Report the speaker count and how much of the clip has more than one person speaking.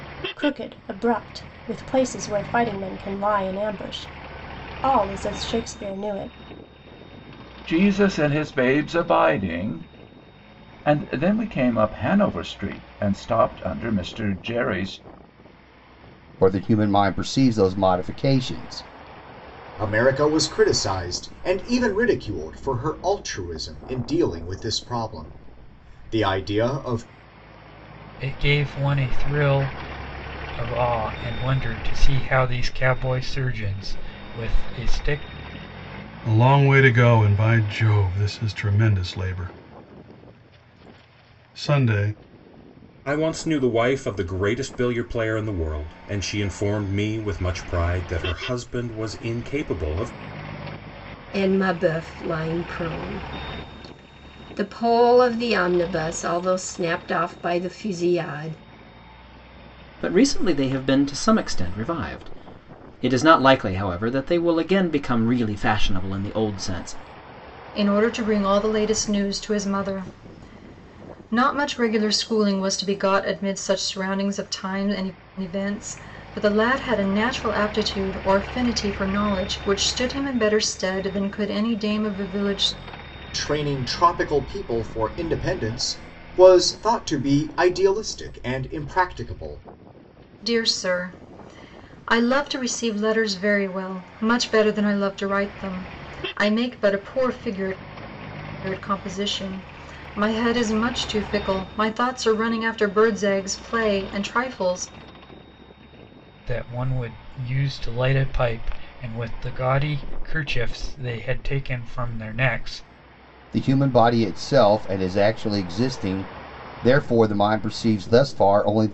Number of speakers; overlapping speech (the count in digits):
10, no overlap